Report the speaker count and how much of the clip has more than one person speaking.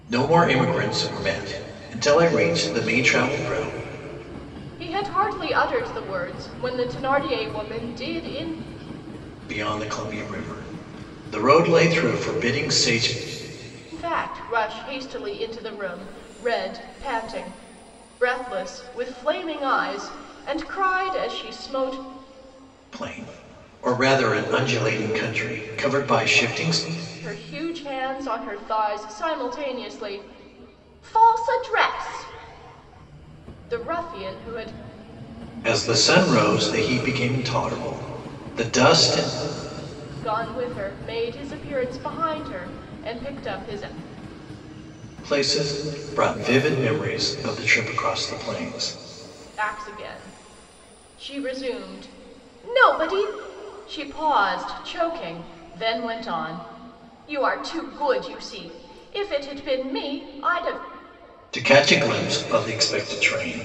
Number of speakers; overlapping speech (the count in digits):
2, no overlap